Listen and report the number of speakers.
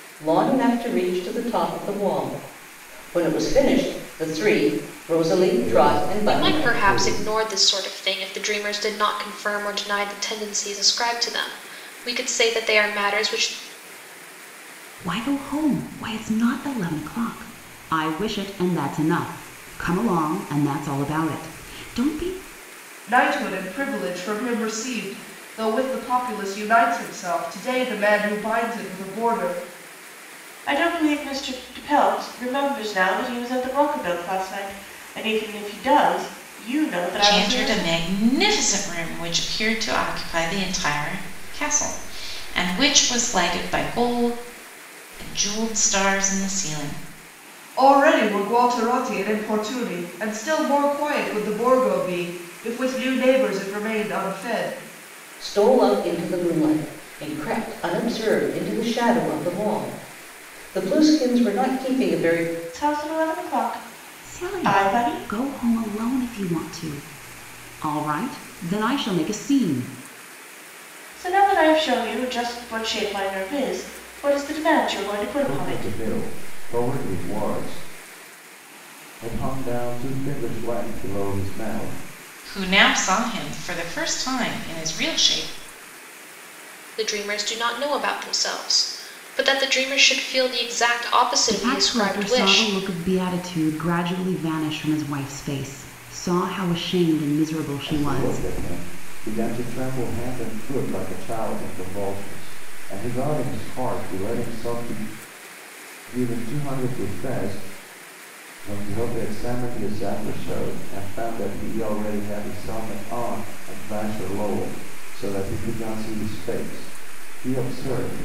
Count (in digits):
7